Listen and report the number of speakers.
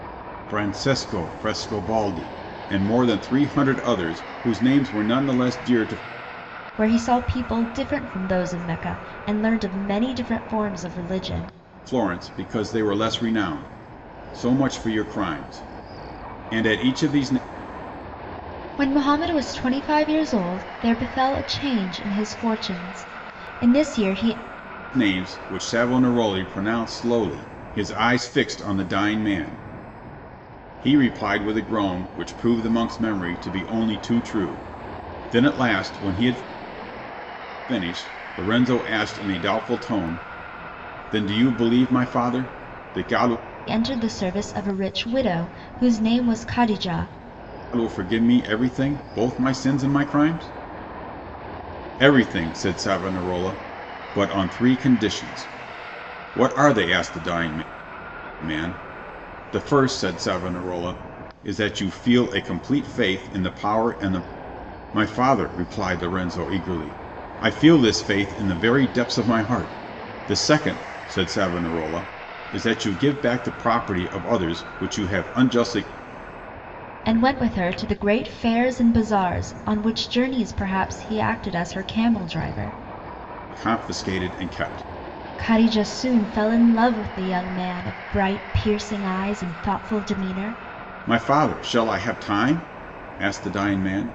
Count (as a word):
two